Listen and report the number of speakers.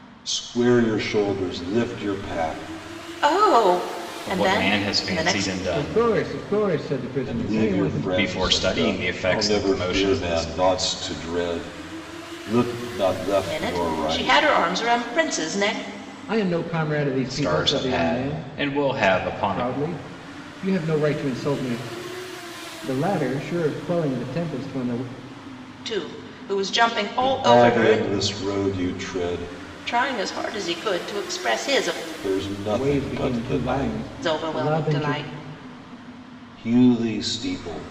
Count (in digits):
4